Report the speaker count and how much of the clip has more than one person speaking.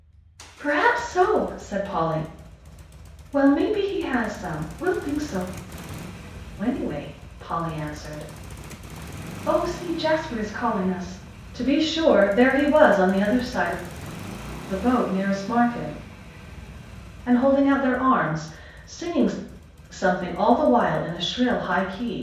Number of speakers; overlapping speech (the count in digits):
1, no overlap